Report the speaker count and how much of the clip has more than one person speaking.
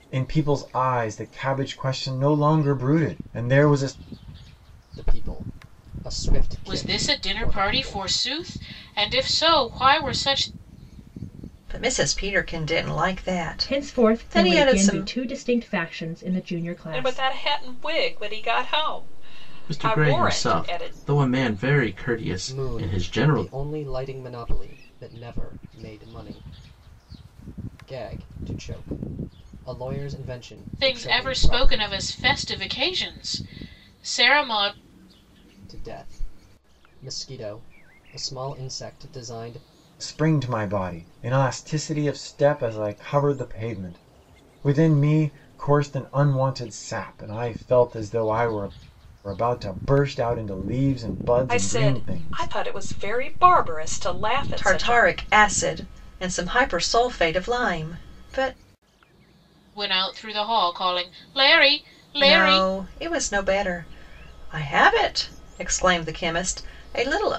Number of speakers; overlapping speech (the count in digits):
7, about 13%